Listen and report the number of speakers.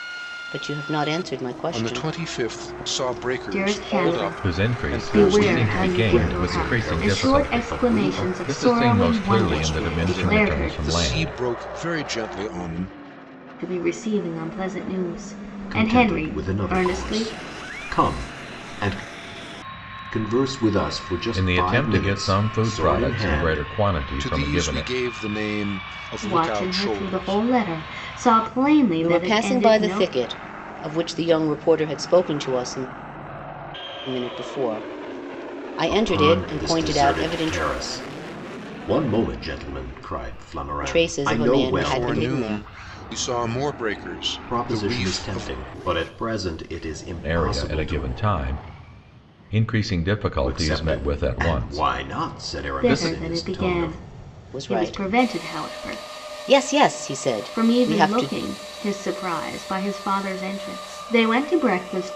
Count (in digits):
5